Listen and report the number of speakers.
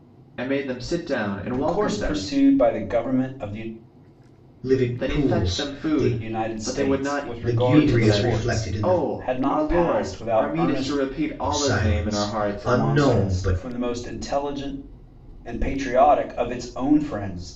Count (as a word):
three